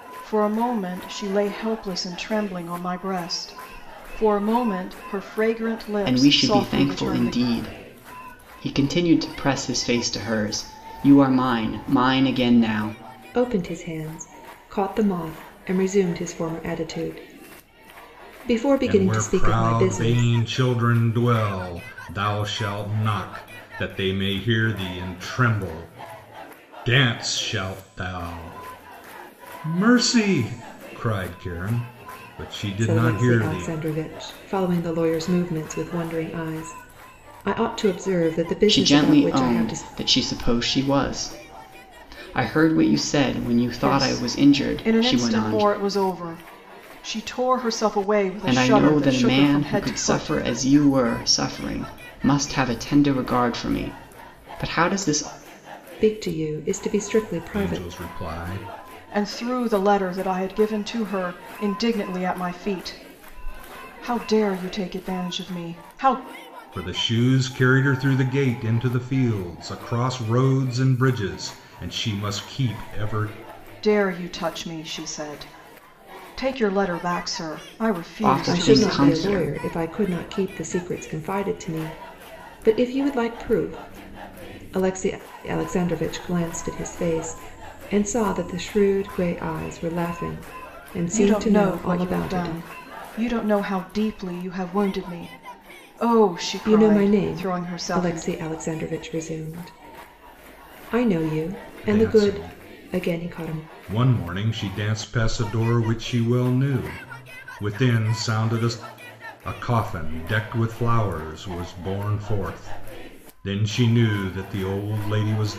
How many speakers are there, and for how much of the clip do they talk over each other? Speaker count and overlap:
4, about 14%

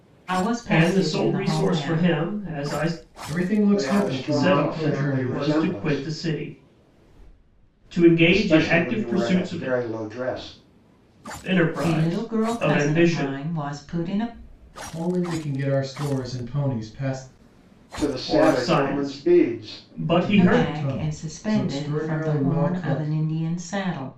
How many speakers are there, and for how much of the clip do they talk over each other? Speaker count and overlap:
4, about 46%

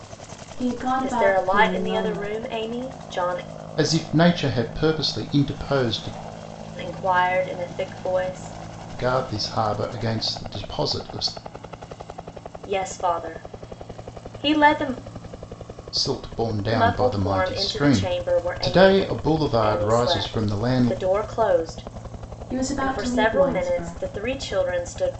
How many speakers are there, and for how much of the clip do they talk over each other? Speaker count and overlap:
3, about 24%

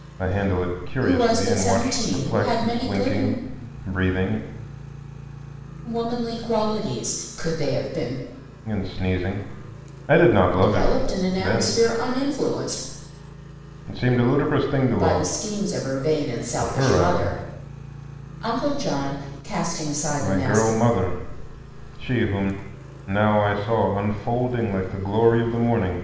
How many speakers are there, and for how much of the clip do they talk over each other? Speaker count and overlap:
2, about 21%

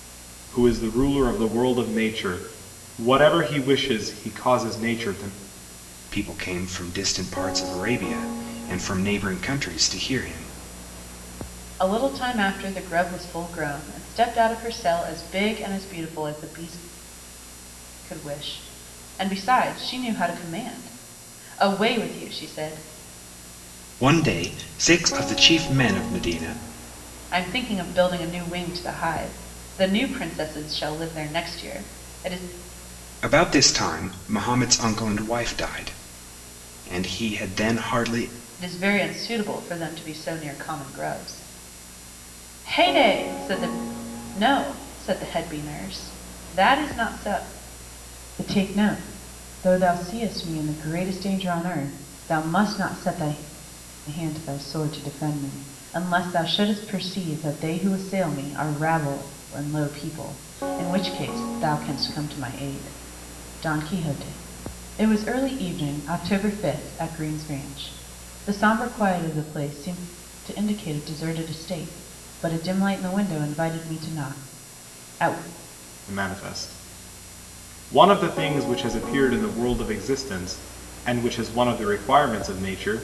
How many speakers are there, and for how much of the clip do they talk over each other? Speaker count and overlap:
3, no overlap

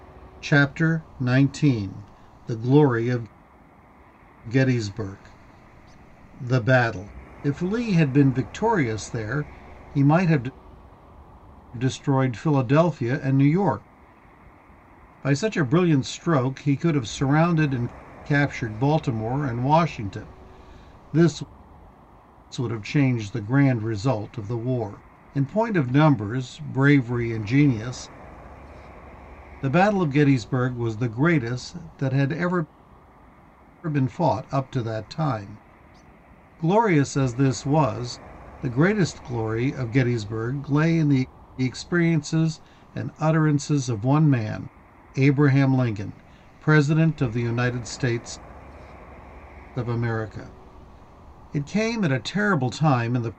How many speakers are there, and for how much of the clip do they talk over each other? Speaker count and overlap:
1, no overlap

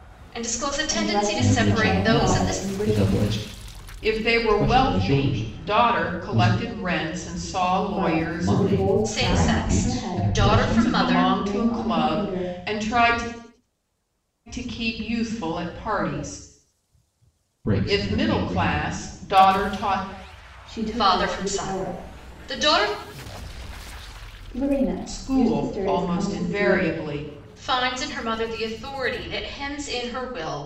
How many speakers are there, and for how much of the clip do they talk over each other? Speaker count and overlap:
4, about 42%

